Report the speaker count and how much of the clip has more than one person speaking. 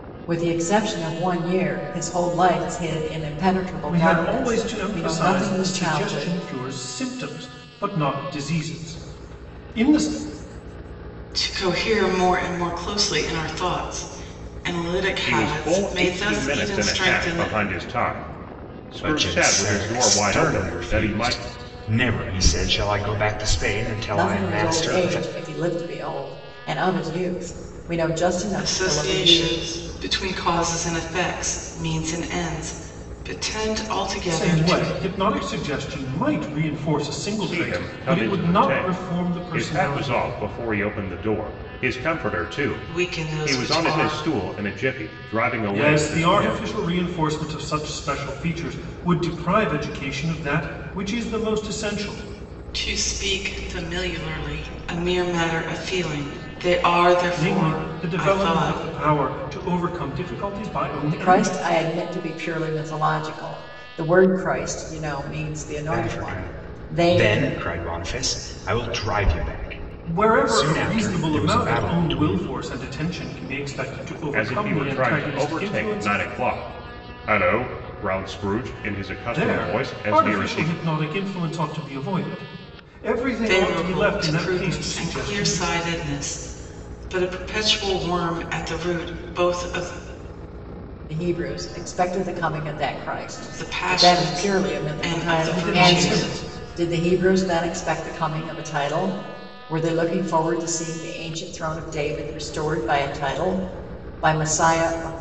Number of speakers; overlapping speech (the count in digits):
5, about 29%